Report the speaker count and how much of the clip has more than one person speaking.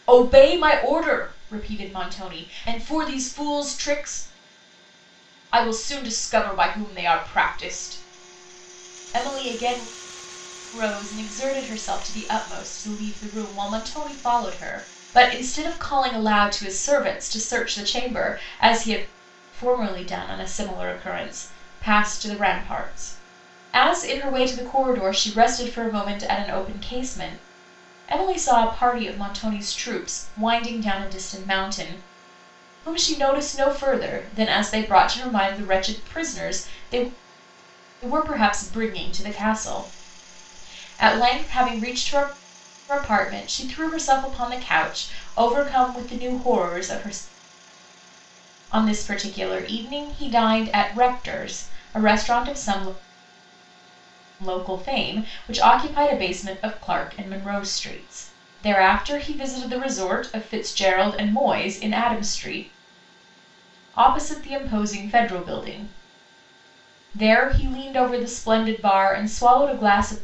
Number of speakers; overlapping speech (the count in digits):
1, no overlap